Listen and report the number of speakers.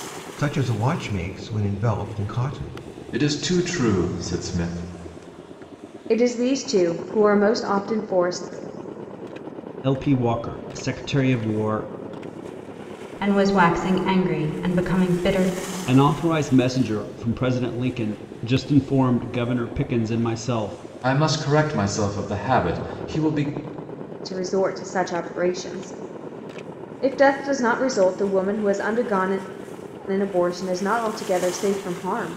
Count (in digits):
5